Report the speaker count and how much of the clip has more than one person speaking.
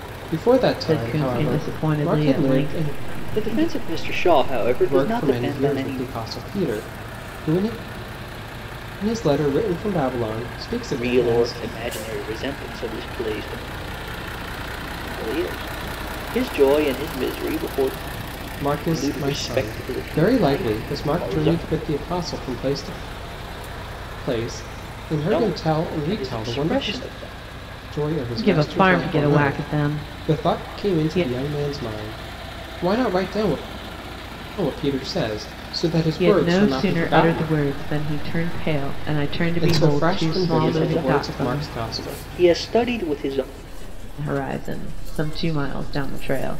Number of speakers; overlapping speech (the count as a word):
four, about 44%